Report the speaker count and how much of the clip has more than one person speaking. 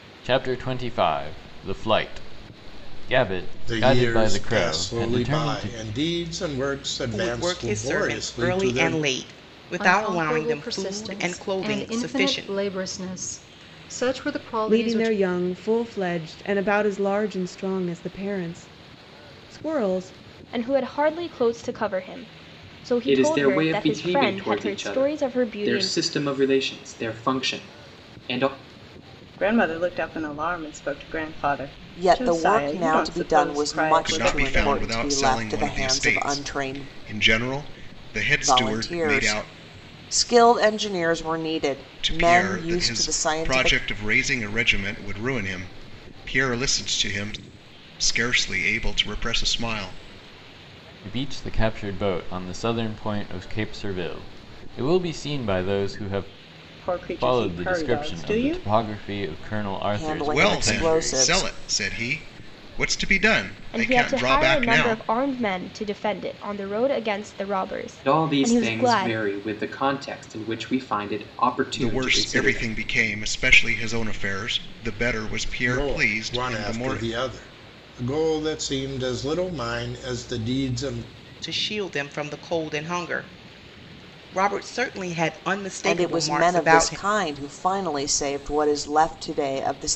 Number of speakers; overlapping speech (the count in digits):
10, about 31%